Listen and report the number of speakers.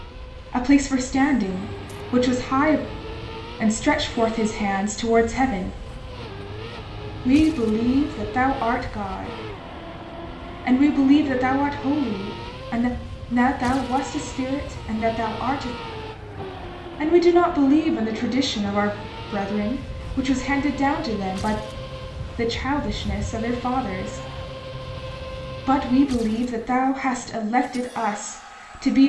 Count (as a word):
one